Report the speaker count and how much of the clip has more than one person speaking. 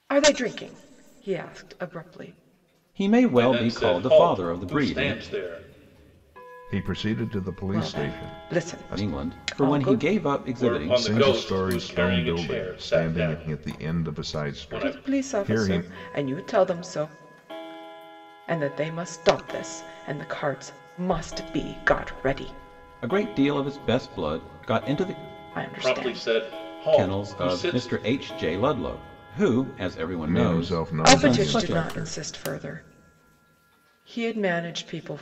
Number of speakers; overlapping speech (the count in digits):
4, about 37%